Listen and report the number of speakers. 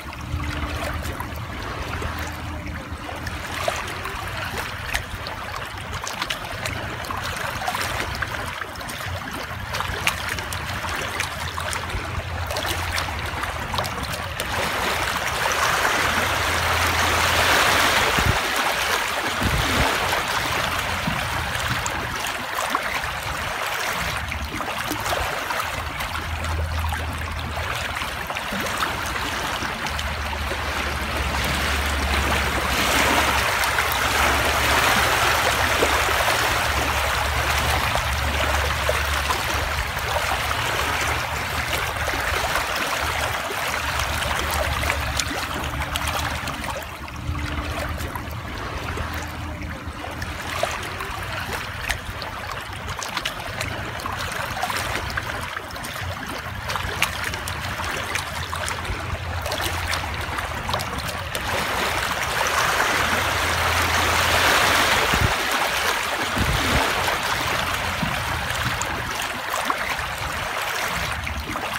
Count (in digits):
0